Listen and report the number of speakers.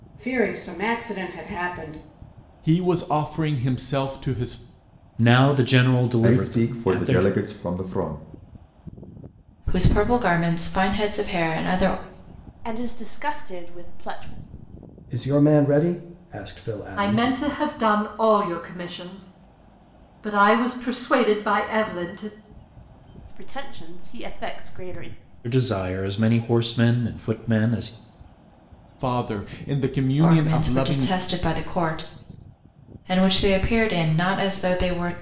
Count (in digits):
8